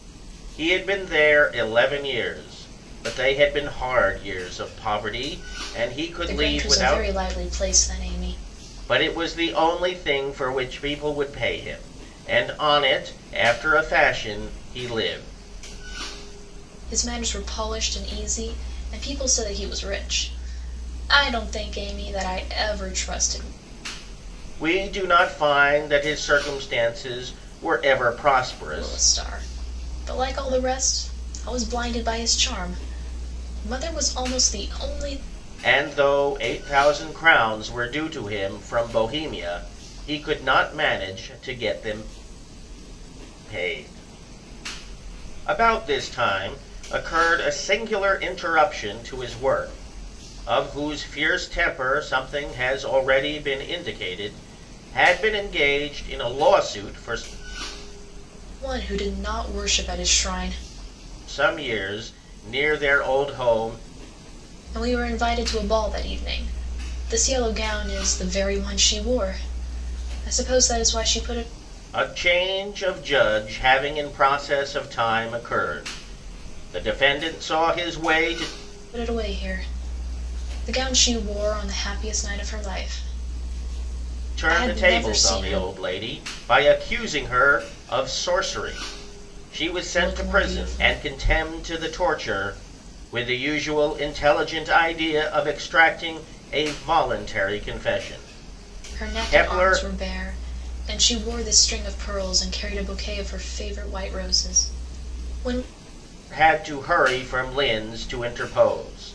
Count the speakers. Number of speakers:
2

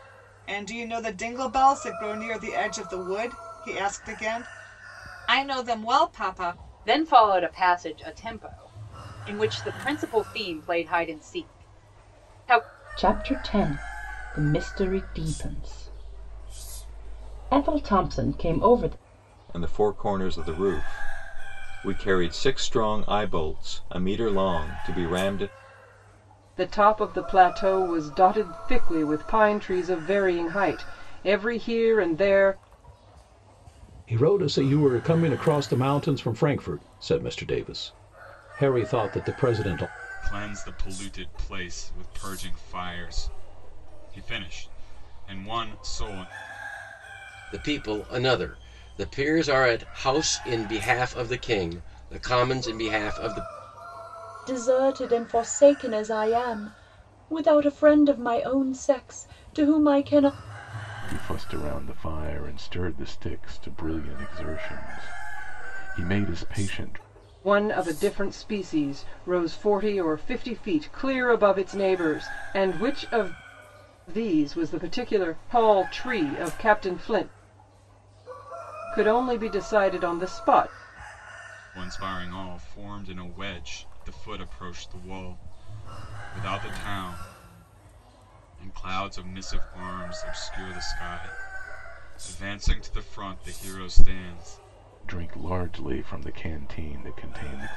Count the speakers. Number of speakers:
10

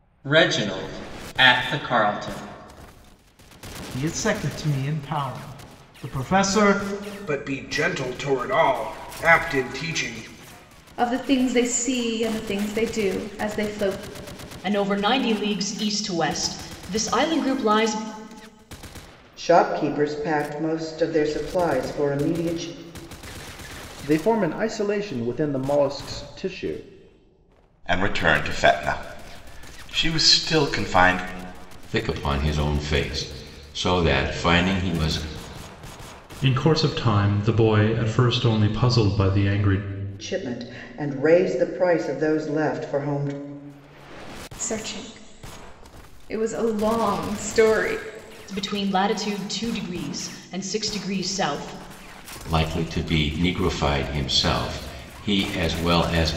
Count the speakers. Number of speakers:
10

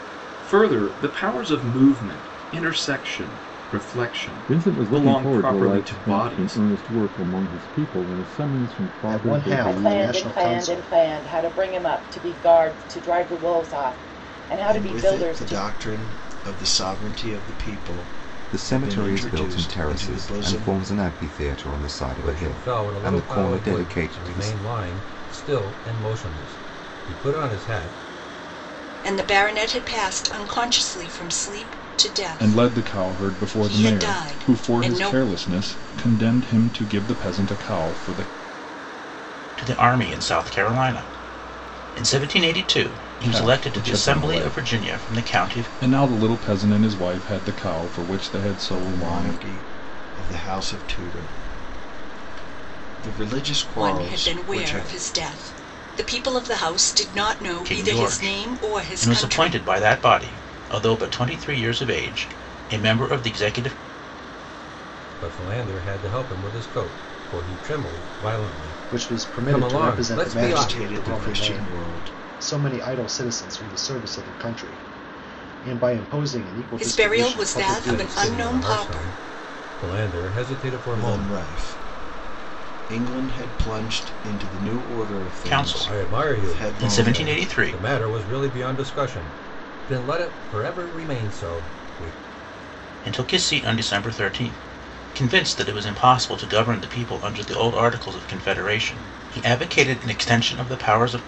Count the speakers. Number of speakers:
10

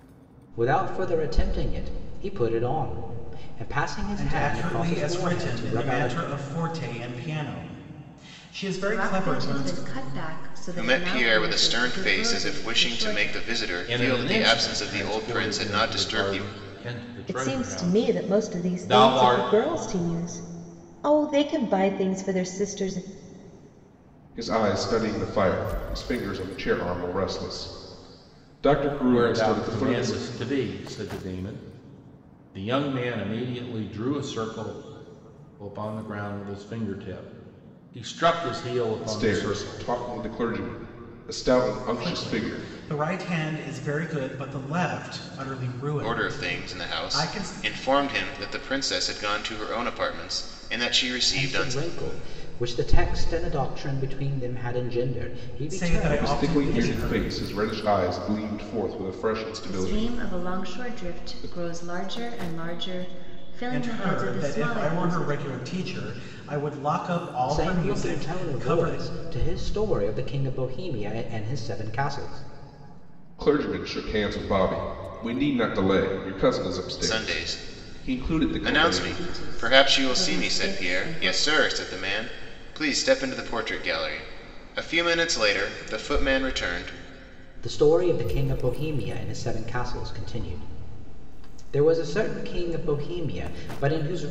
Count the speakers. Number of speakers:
7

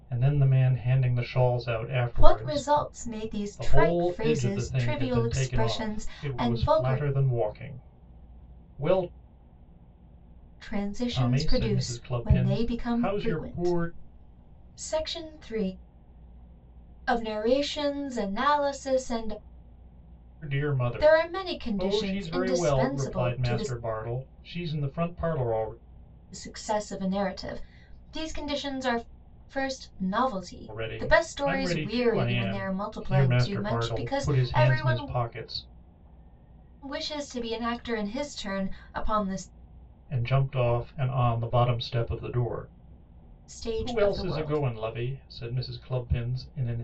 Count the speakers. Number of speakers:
2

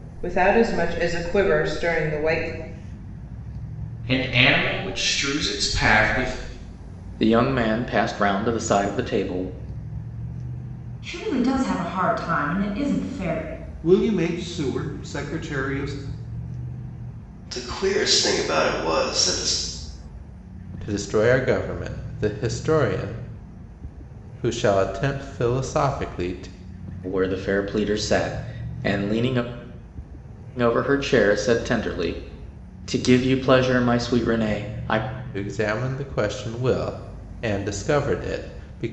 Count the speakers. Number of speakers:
7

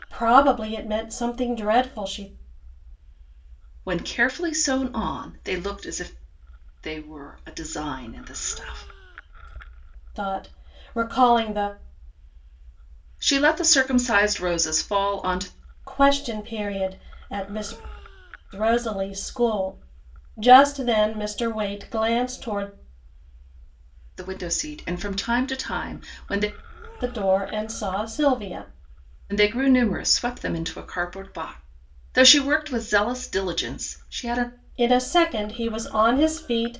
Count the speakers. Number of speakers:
2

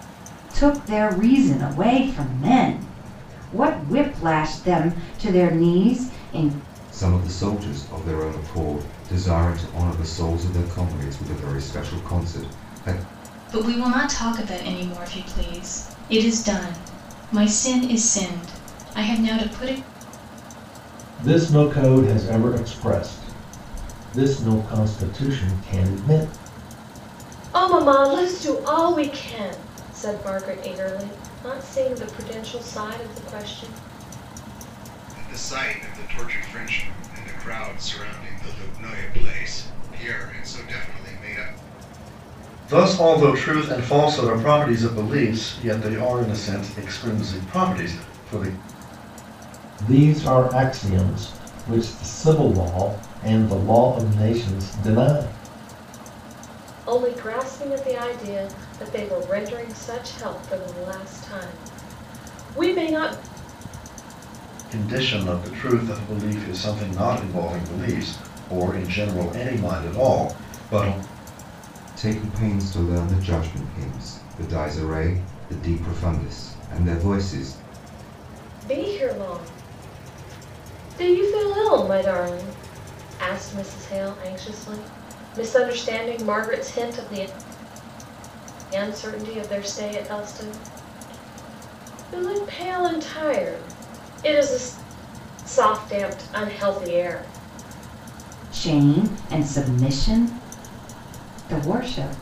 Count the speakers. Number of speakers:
7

